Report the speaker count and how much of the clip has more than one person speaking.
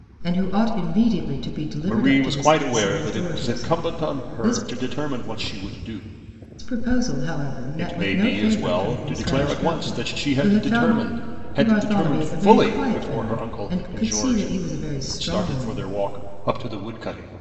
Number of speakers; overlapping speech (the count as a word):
two, about 55%